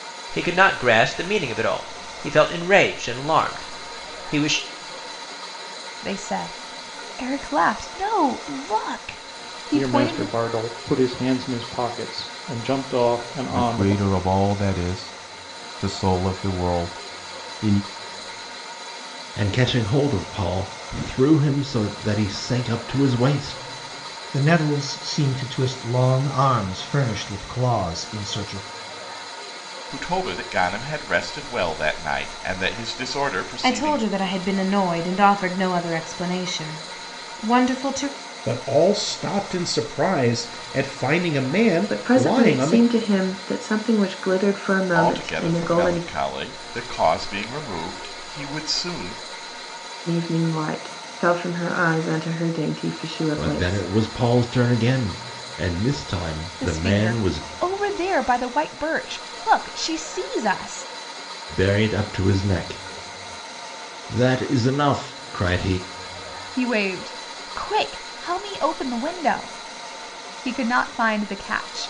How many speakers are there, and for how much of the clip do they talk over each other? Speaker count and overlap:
ten, about 8%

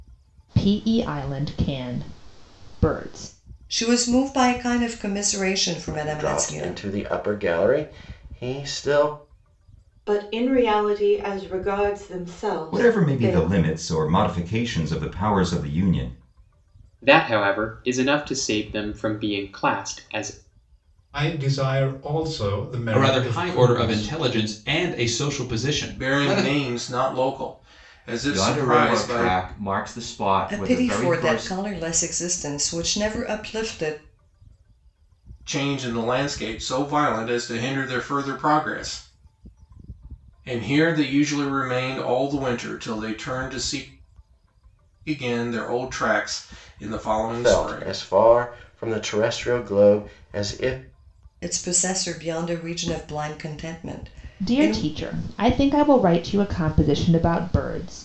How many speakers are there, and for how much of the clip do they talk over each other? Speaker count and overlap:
ten, about 12%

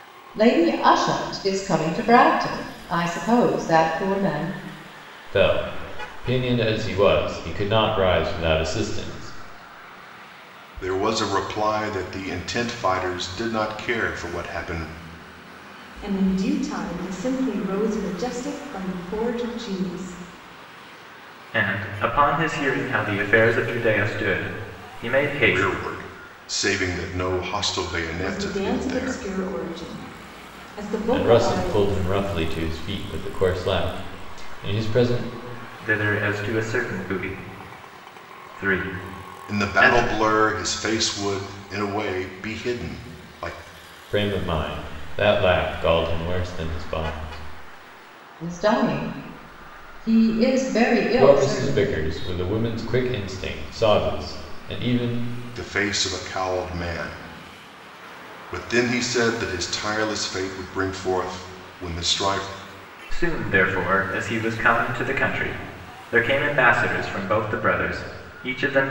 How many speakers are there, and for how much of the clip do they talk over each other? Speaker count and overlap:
five, about 6%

